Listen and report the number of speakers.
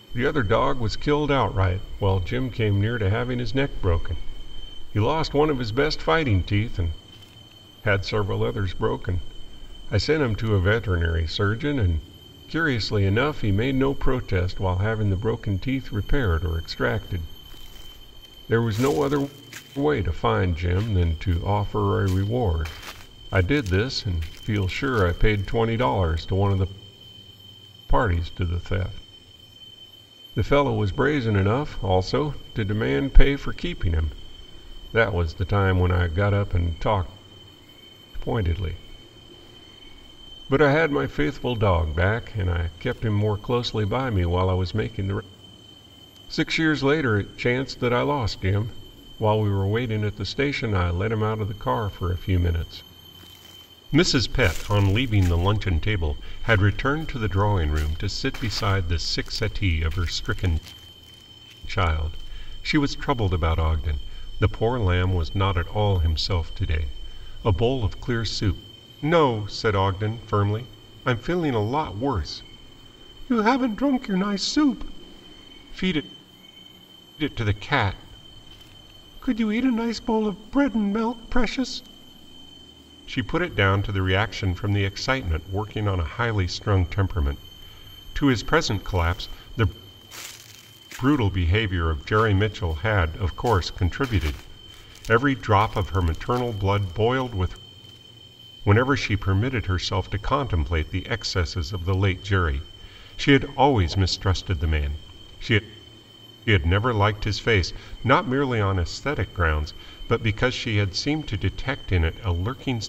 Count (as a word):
one